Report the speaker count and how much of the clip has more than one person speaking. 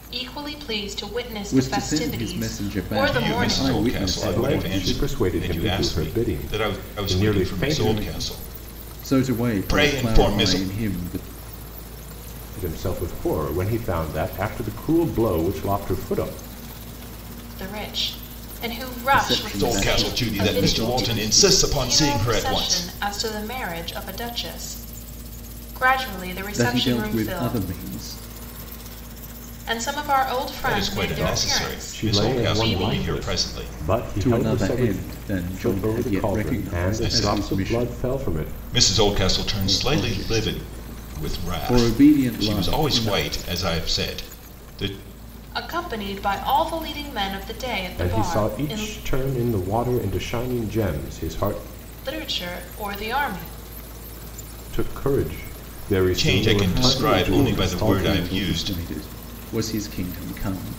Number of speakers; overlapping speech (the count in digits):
4, about 46%